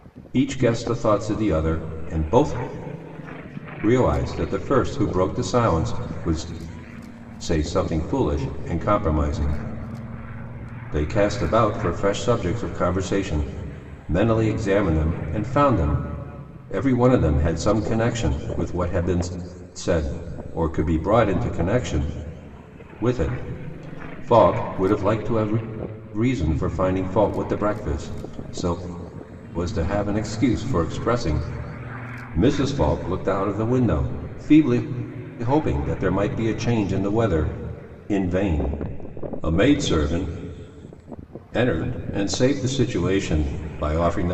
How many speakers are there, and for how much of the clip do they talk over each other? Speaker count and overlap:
one, no overlap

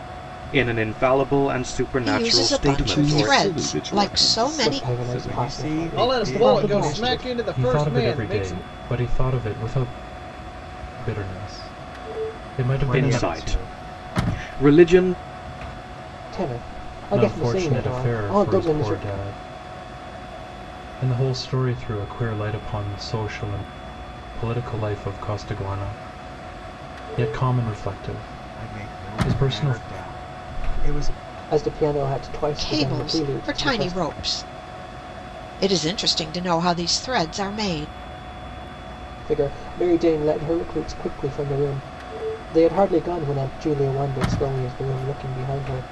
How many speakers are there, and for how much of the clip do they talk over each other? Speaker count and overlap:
seven, about 27%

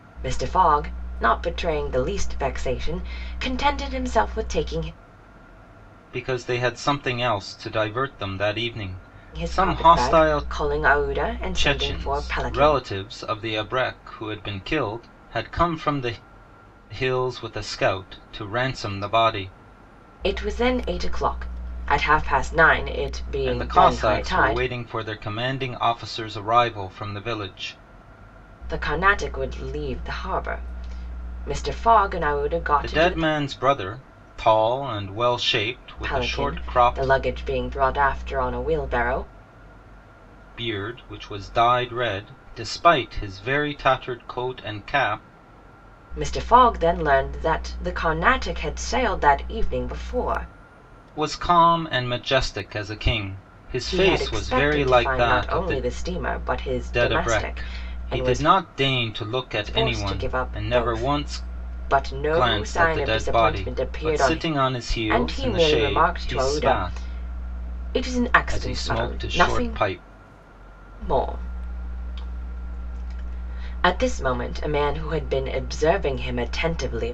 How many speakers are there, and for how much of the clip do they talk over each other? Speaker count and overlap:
two, about 21%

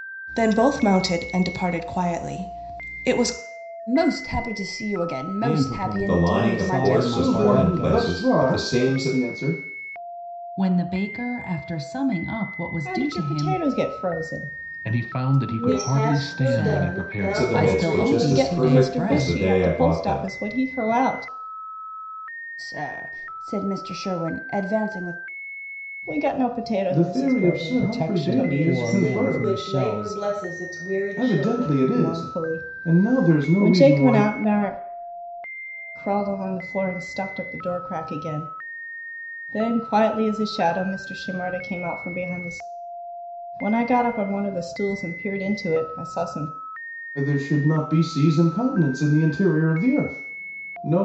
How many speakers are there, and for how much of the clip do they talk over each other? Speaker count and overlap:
nine, about 32%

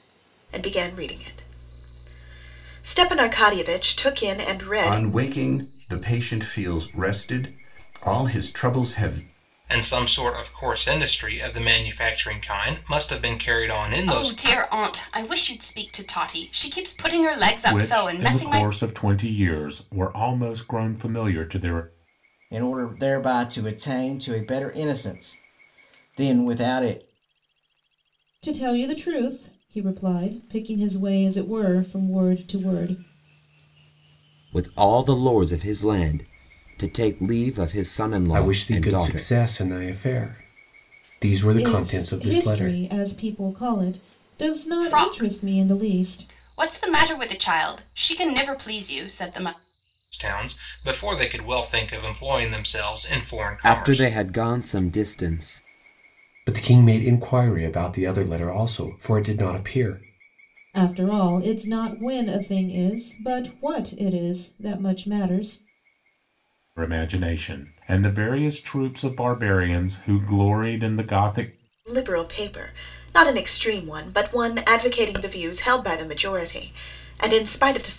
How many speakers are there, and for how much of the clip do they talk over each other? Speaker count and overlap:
nine, about 8%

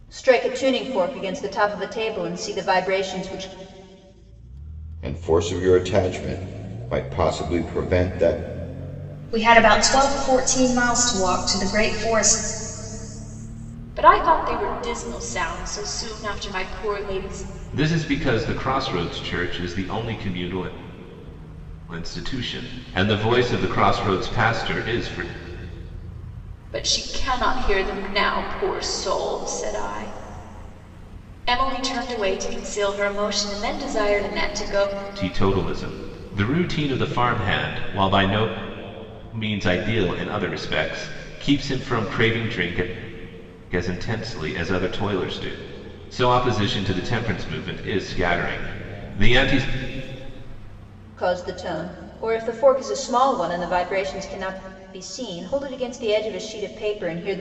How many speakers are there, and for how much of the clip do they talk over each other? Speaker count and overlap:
five, no overlap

